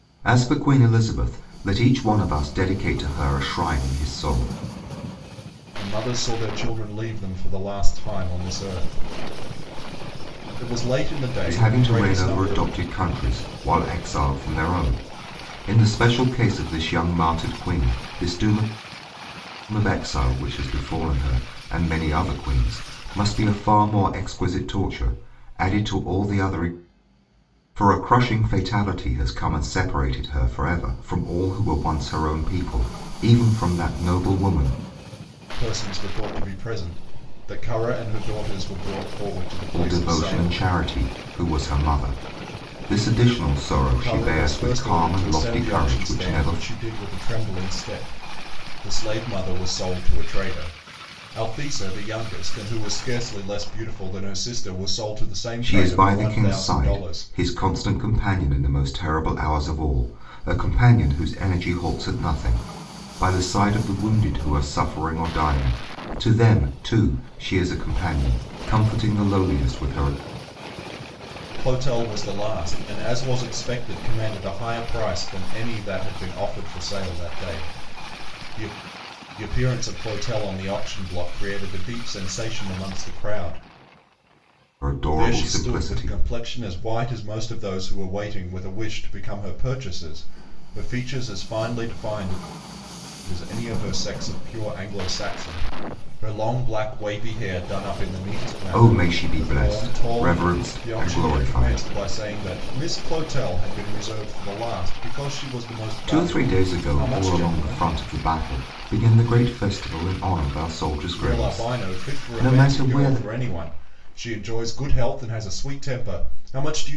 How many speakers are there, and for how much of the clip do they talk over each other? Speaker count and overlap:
two, about 12%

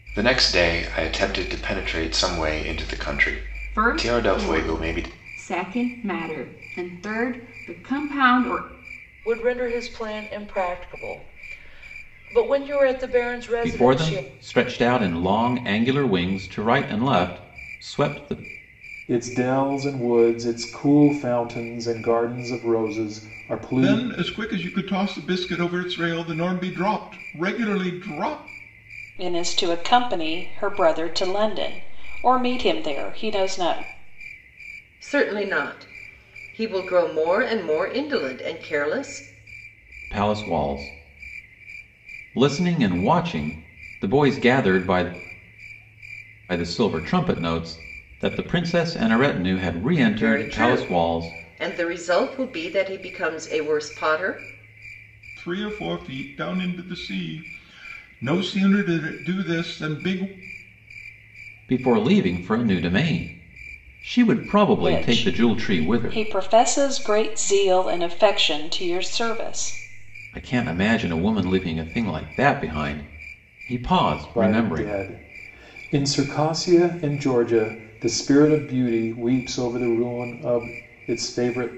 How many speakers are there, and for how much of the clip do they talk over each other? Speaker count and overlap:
eight, about 7%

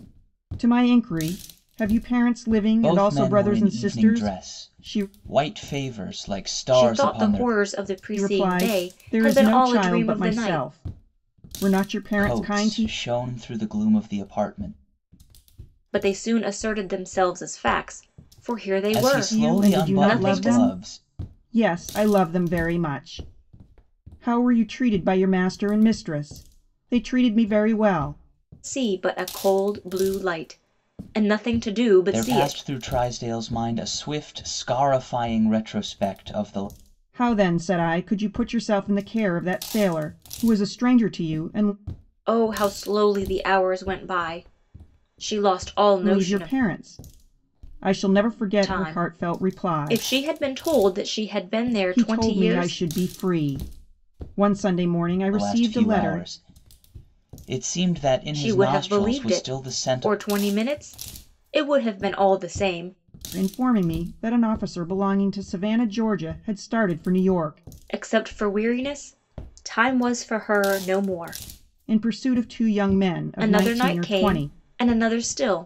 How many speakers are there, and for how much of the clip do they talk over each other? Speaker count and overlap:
three, about 21%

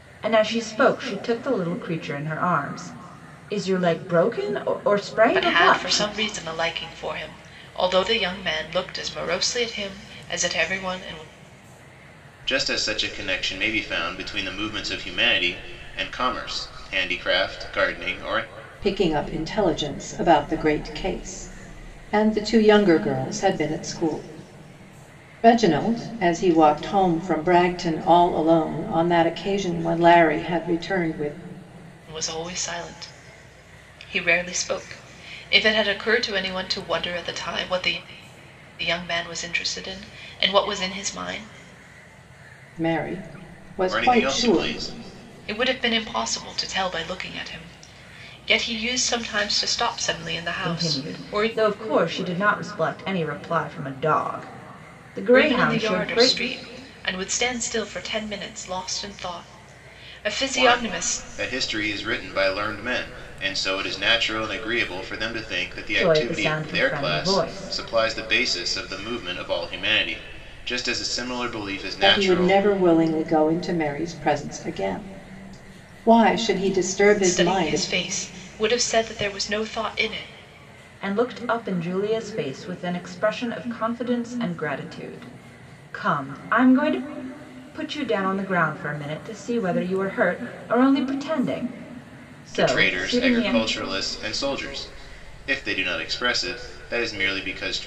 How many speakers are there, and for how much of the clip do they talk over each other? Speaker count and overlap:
four, about 9%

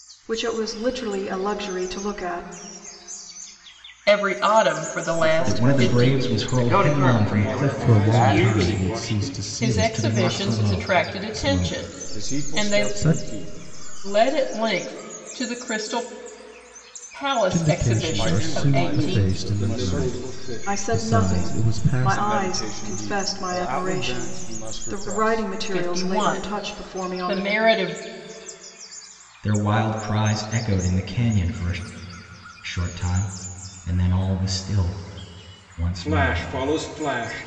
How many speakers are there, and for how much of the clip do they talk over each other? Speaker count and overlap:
seven, about 48%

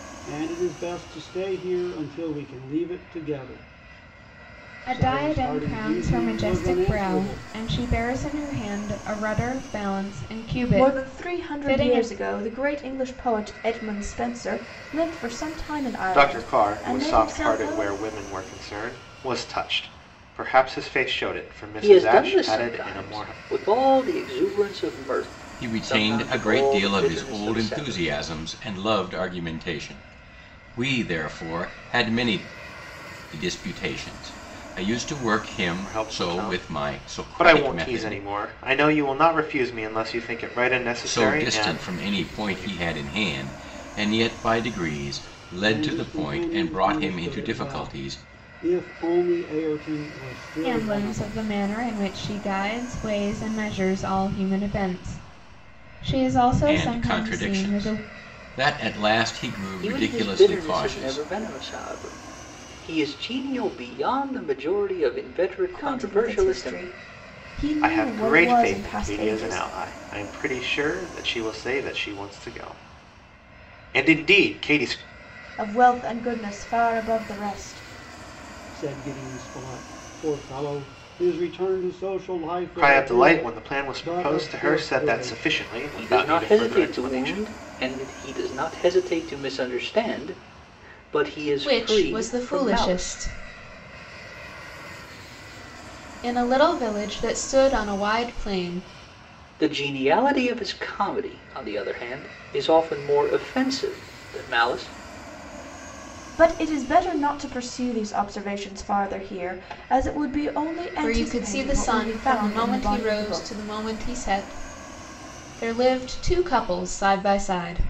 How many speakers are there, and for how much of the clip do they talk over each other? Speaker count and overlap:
six, about 28%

